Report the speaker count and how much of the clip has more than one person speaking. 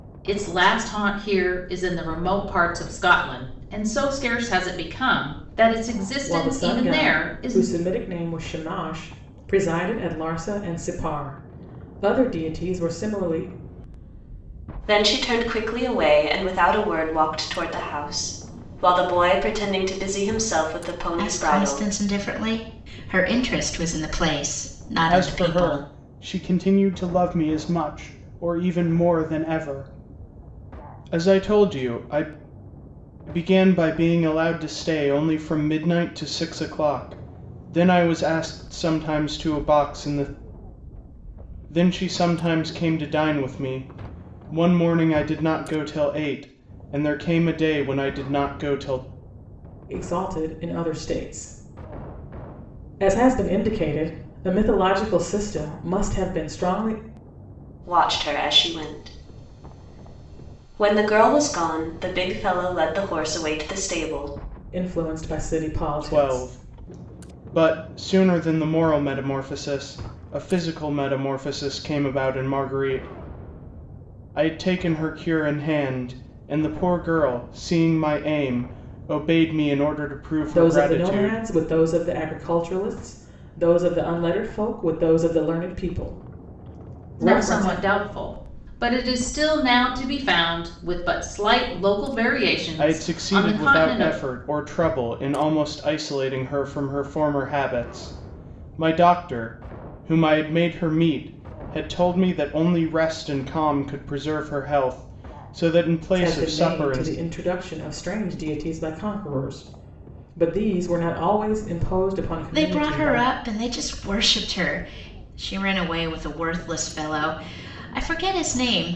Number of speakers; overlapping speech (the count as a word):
five, about 7%